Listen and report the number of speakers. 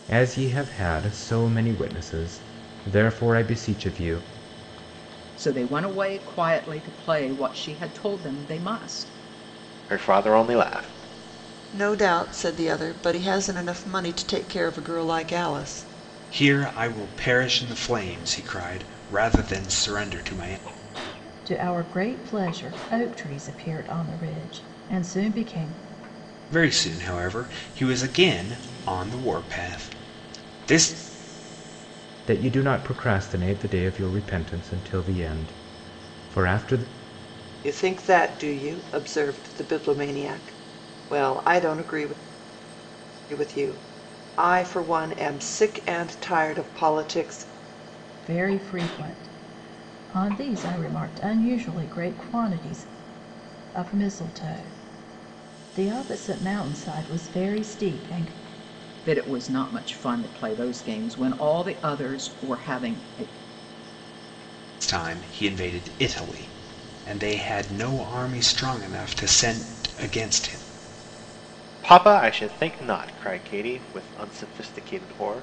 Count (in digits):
6